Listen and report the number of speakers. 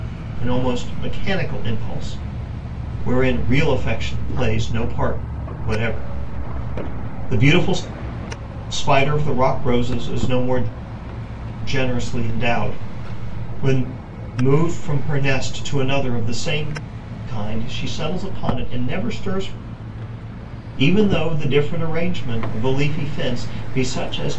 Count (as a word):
one